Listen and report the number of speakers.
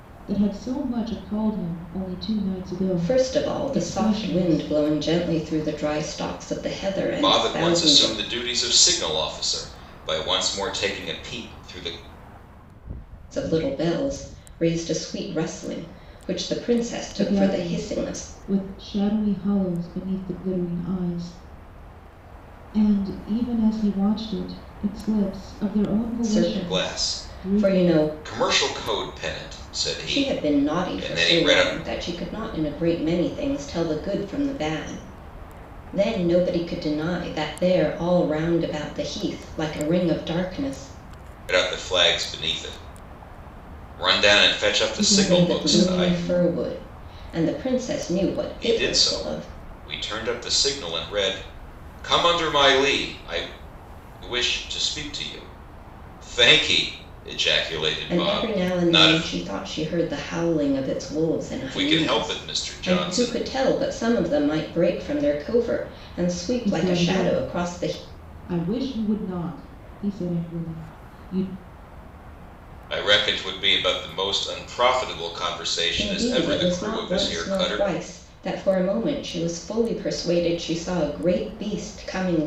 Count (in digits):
3